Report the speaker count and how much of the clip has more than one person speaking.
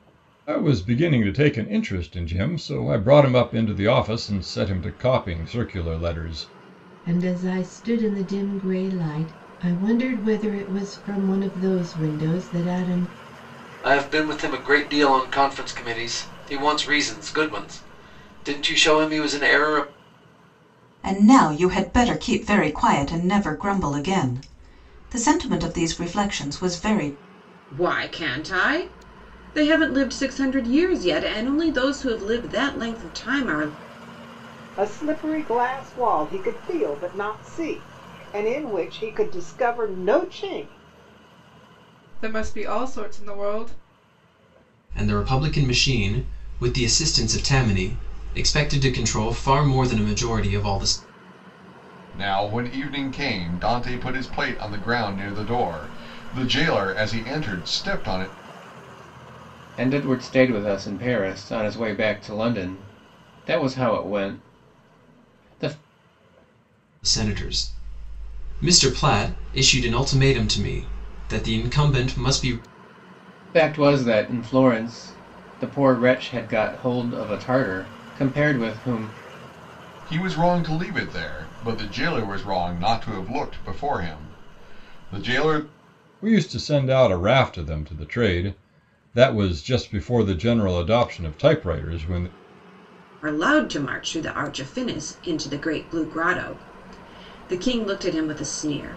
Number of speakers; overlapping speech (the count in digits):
10, no overlap